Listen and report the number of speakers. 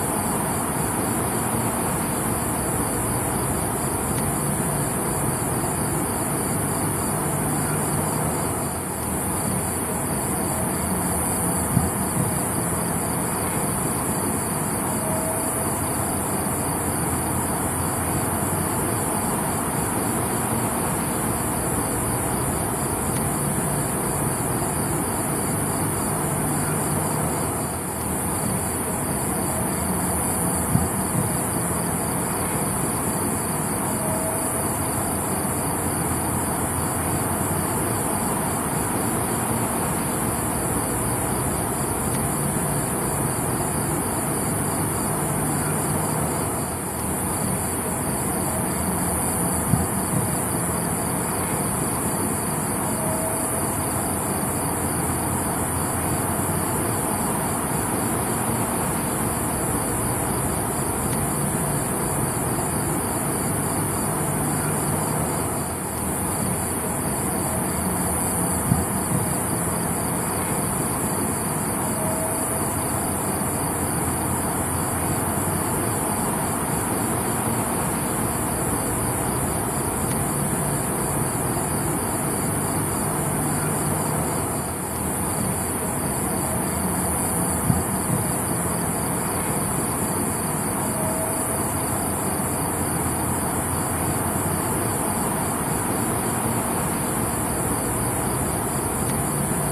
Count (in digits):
0